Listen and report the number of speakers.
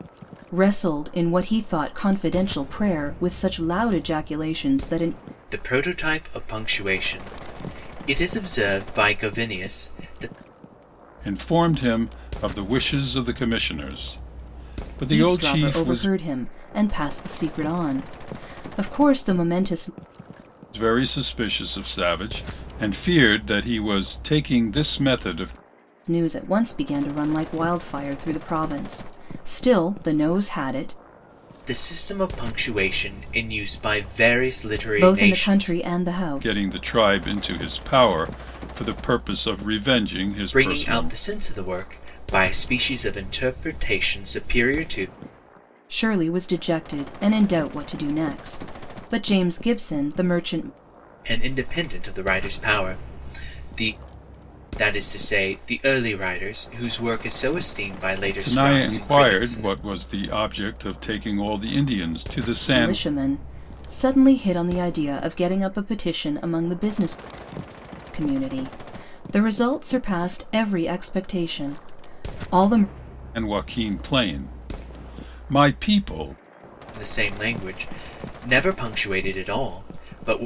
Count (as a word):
three